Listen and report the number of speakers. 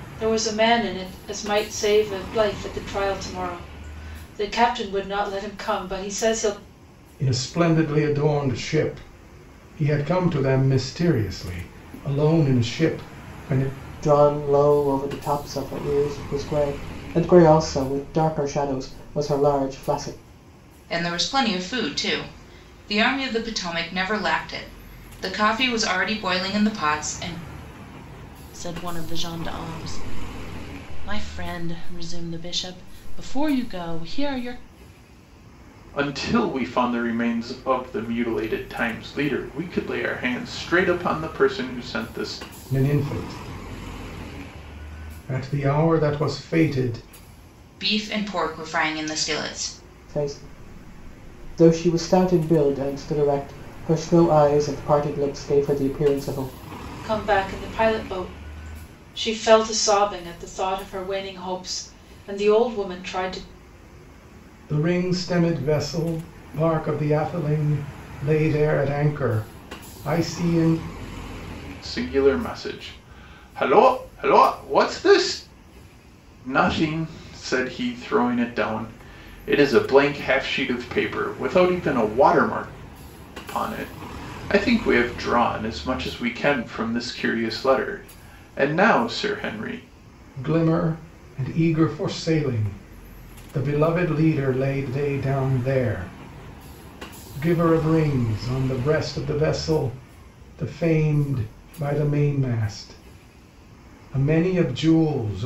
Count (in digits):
6